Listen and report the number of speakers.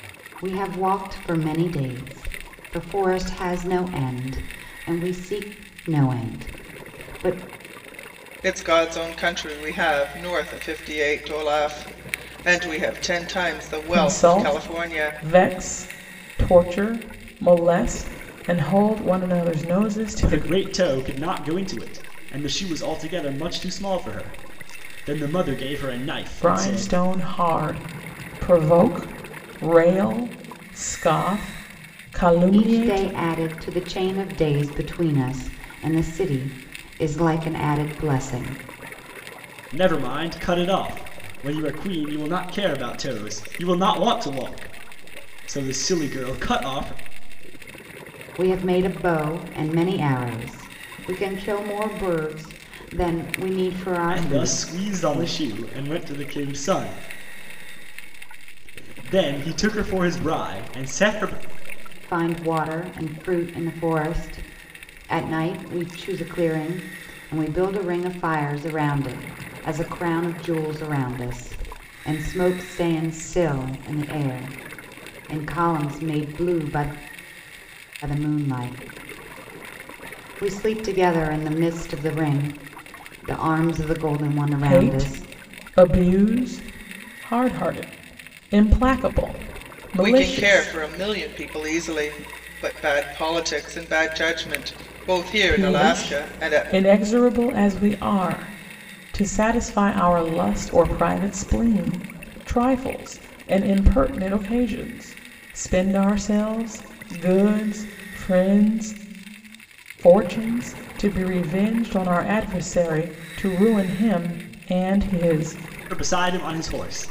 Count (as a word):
four